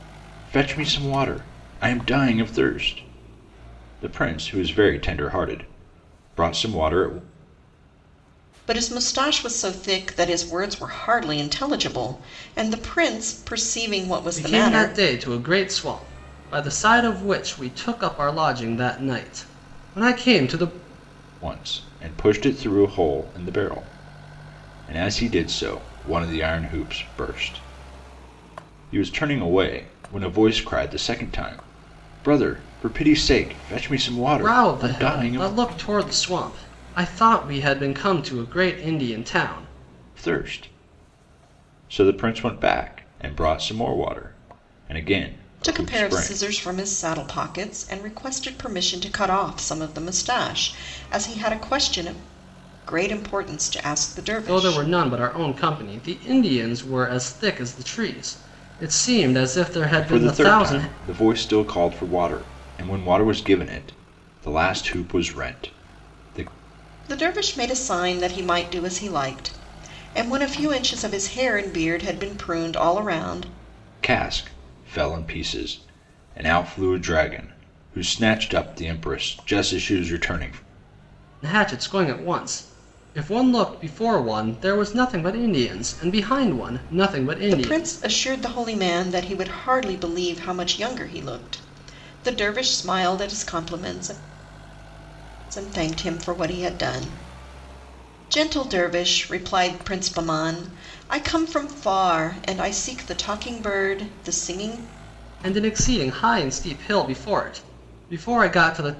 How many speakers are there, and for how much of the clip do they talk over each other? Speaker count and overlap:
3, about 4%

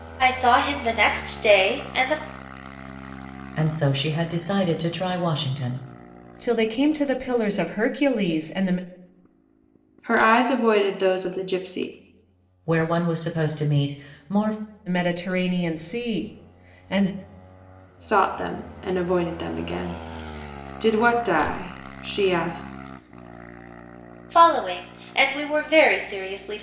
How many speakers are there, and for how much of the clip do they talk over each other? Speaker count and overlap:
4, no overlap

